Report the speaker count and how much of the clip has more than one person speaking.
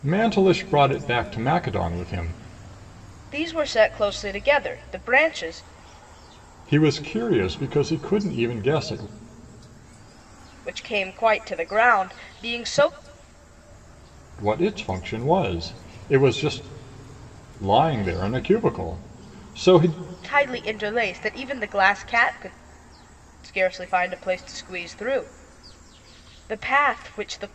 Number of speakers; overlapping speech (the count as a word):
two, no overlap